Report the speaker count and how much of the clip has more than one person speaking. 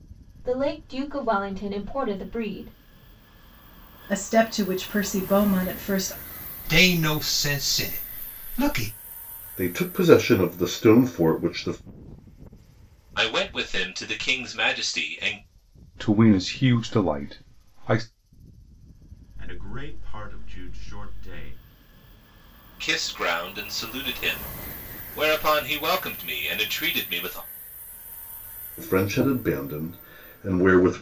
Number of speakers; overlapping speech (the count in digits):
7, no overlap